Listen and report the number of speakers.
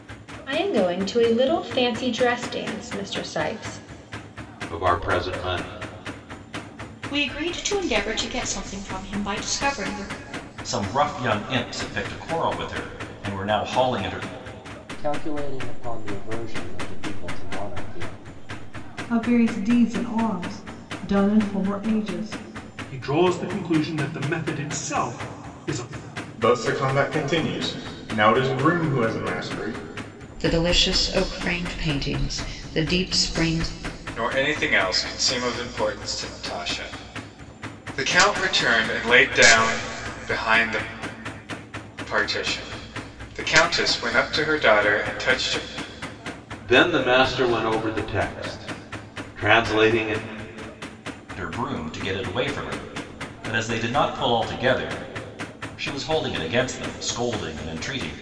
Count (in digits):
10